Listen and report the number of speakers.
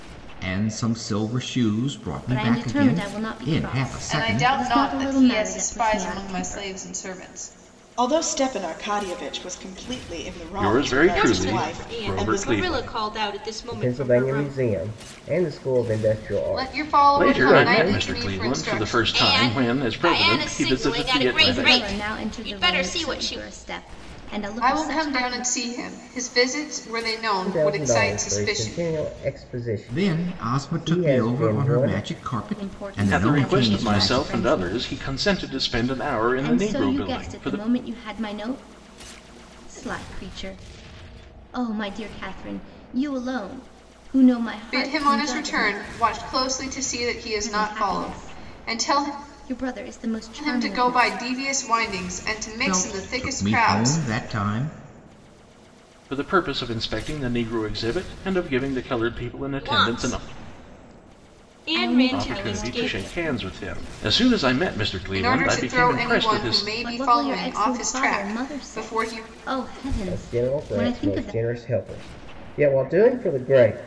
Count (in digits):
7